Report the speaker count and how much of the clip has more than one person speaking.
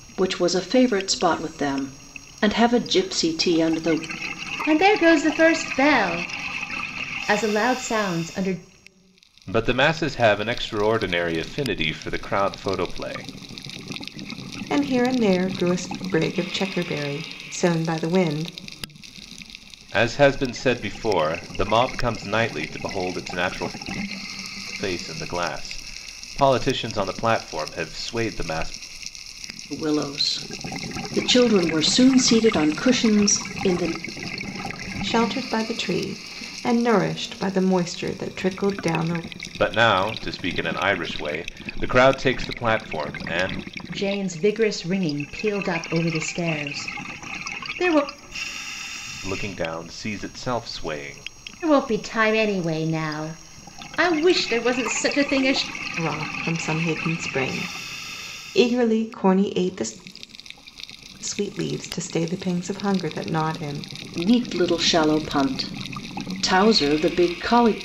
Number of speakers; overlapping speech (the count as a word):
four, no overlap